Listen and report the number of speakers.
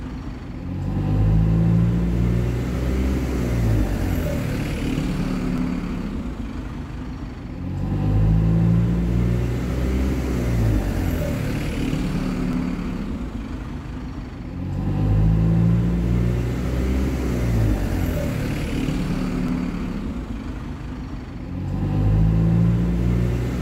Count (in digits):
0